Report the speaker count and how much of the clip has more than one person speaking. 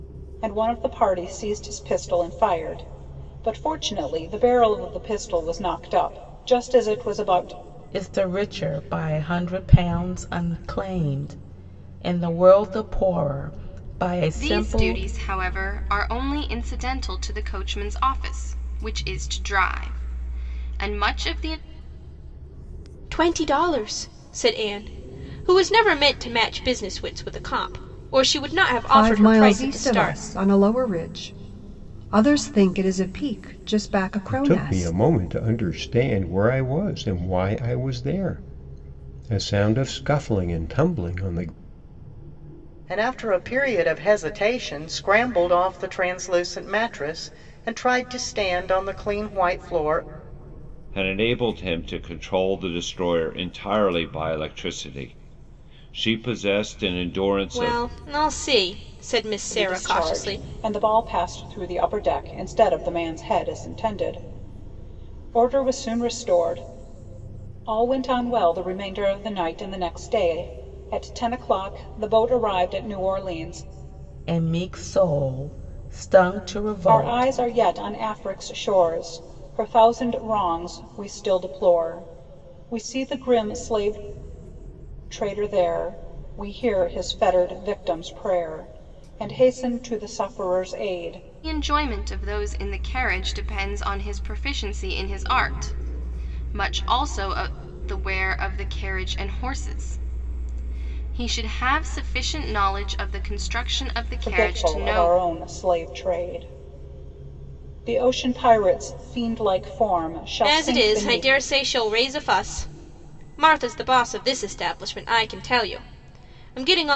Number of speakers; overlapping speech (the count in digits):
8, about 6%